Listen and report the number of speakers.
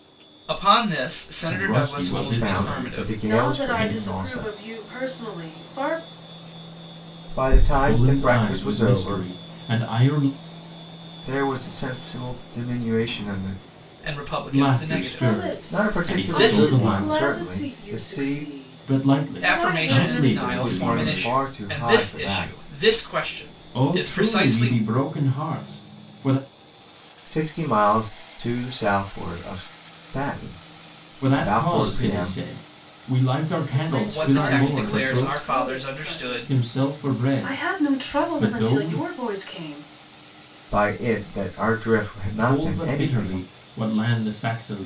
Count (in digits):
4